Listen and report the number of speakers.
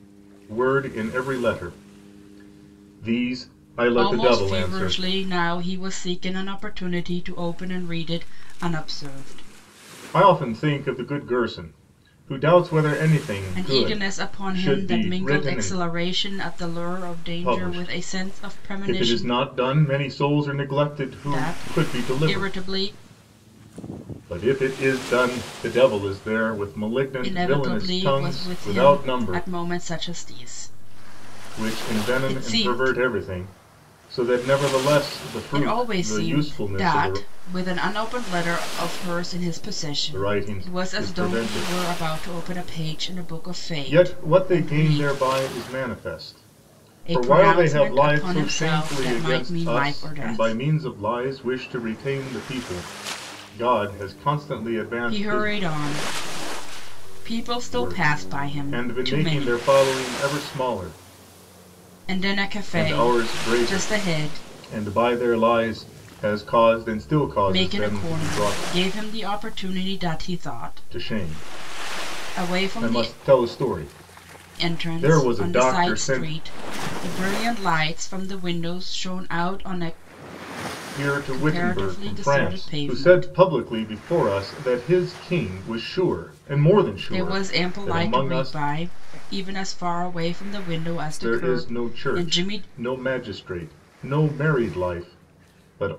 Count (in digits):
2